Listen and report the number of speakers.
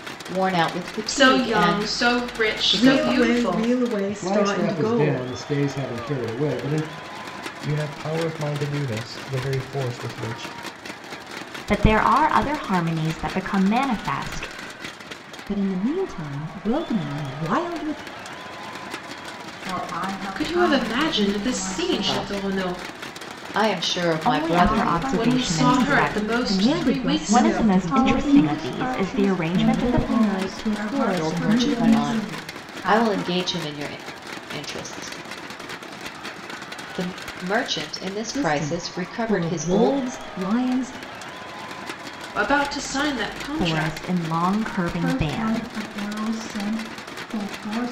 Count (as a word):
eight